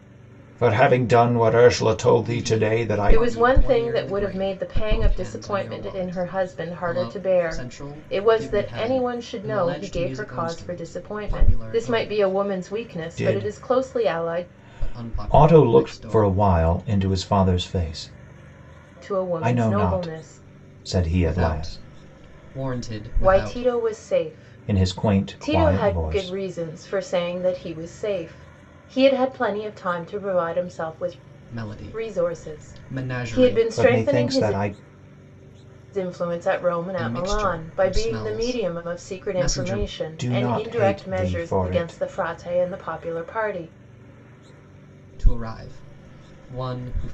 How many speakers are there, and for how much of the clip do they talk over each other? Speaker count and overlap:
three, about 50%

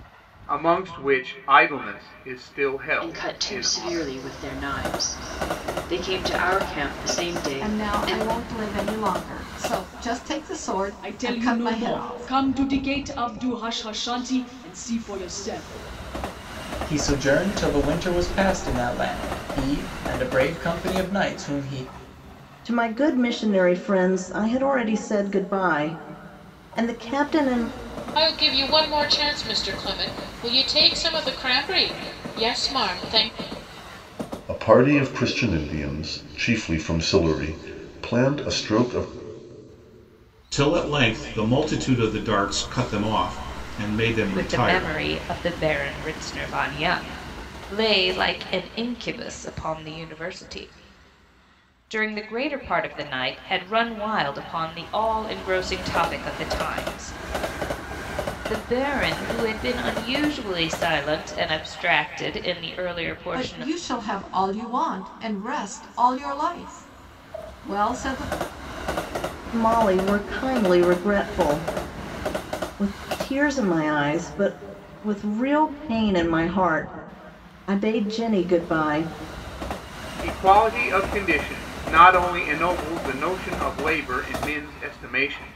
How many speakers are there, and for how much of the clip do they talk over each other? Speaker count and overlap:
ten, about 5%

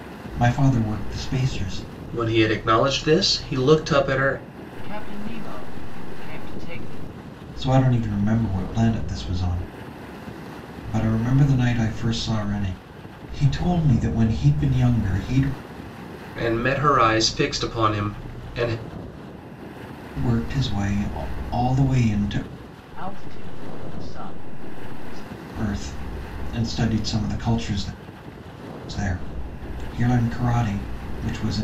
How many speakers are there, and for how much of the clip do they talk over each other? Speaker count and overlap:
three, no overlap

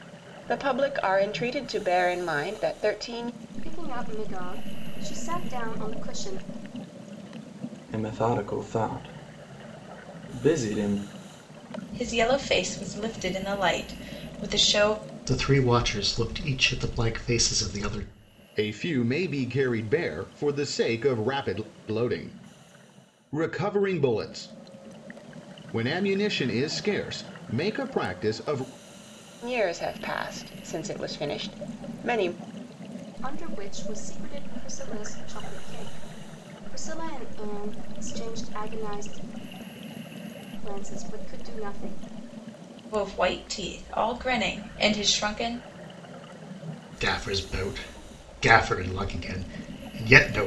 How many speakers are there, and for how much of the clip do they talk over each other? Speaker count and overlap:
six, no overlap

